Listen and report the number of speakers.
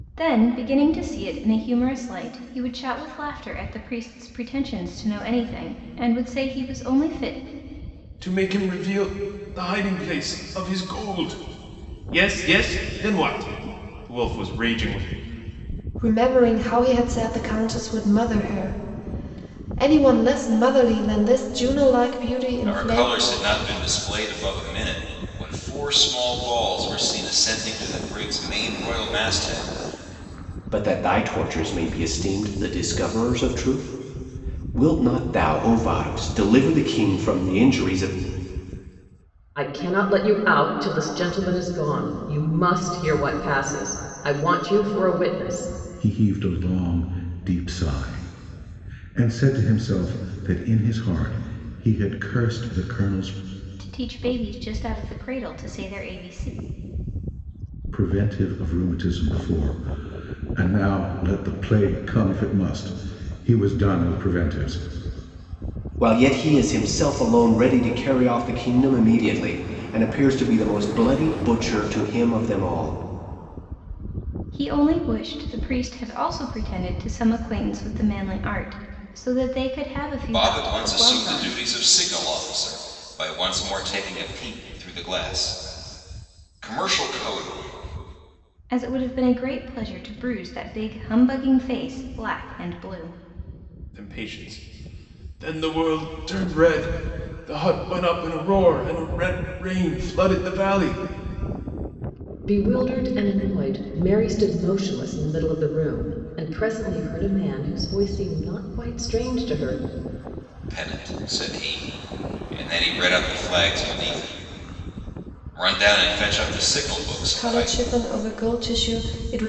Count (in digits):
7